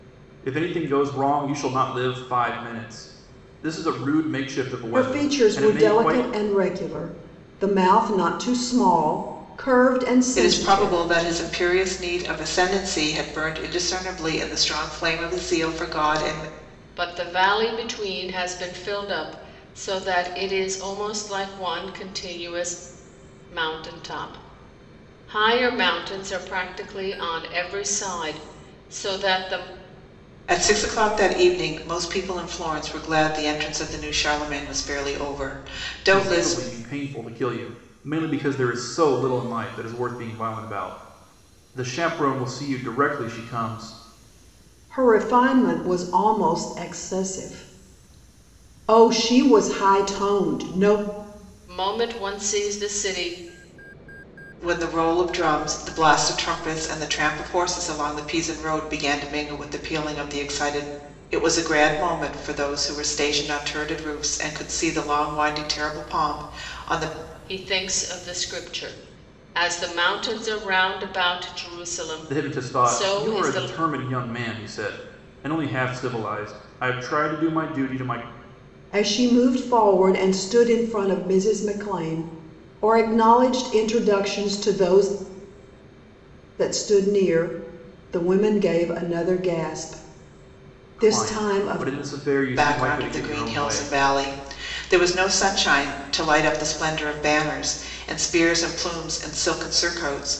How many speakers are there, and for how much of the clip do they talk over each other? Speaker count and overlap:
4, about 7%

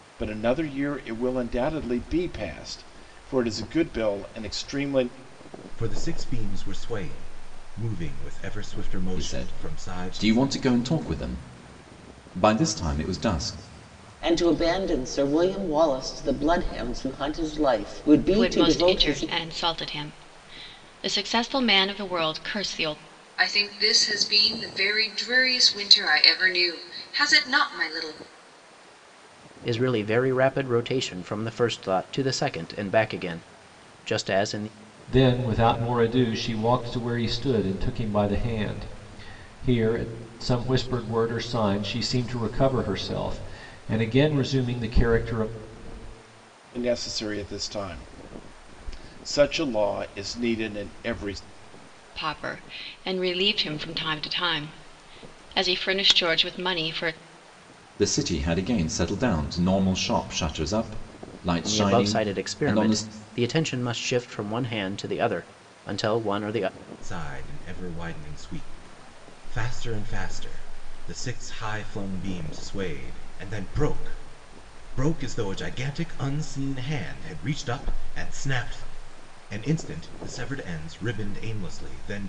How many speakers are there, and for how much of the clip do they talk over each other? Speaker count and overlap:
8, about 5%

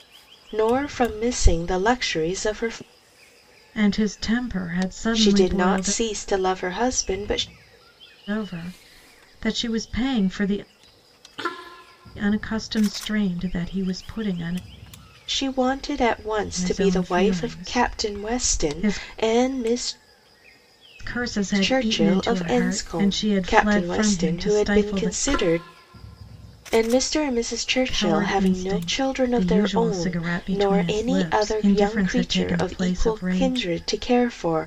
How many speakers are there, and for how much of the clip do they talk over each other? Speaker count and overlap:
2, about 36%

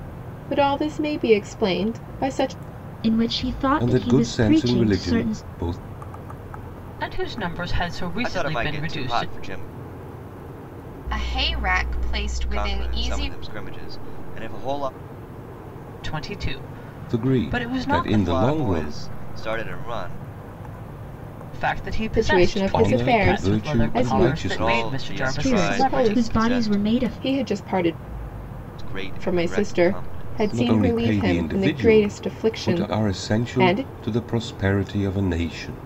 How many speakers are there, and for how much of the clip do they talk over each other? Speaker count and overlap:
6, about 44%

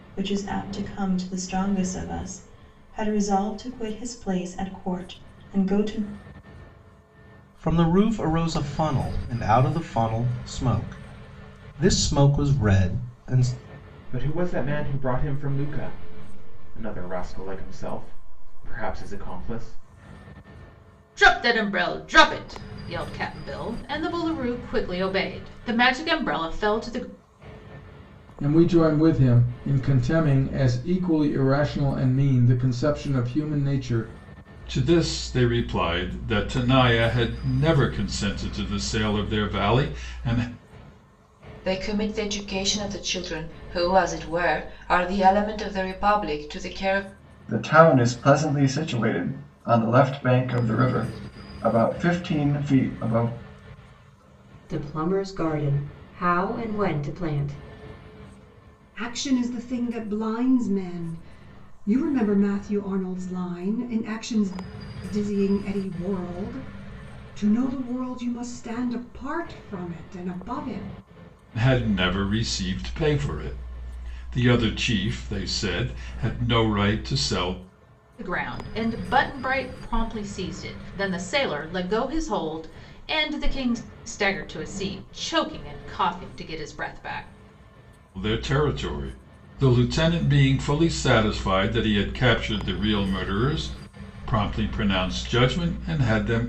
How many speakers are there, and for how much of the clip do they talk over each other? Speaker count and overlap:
10, no overlap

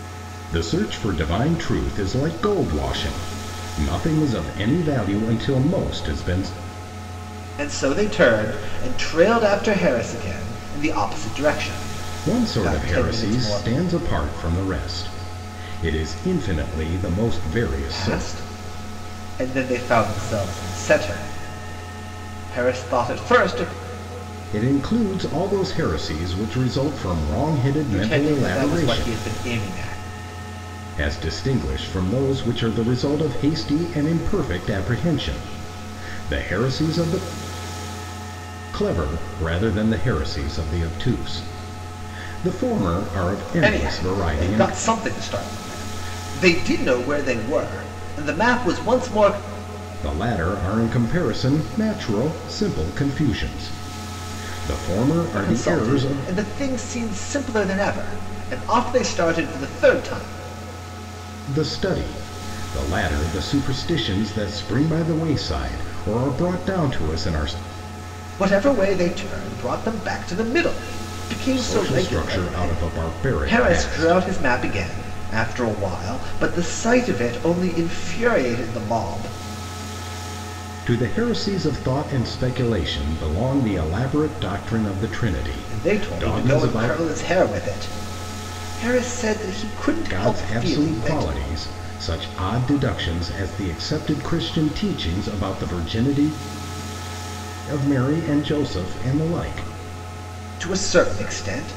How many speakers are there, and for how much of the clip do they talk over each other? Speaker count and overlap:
2, about 10%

